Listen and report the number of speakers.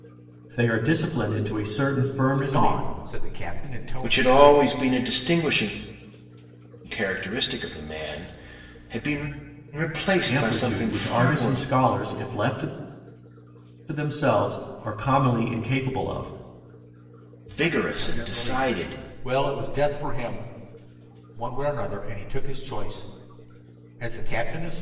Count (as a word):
three